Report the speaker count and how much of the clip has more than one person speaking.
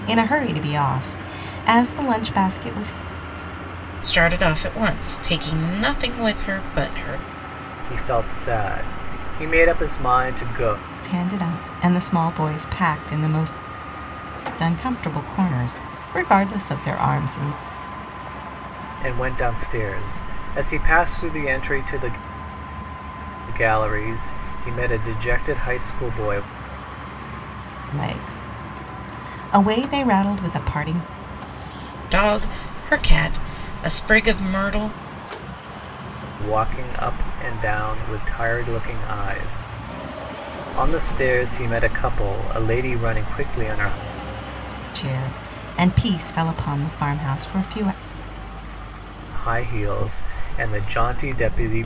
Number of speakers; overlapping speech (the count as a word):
three, no overlap